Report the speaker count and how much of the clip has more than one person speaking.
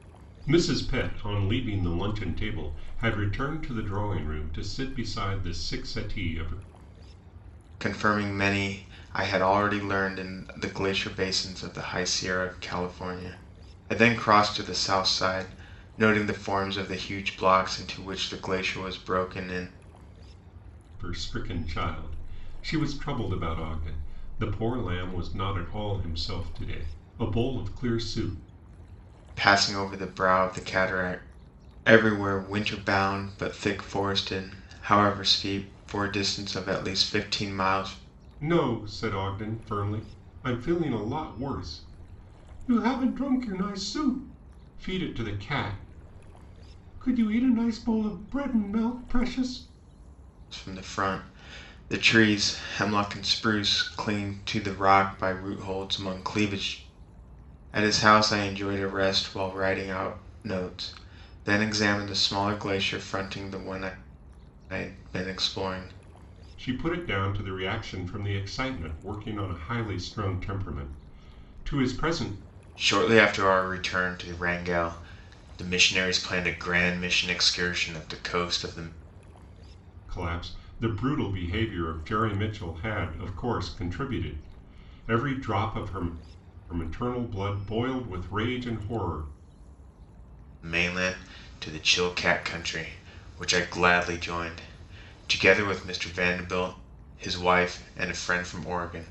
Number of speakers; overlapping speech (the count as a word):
two, no overlap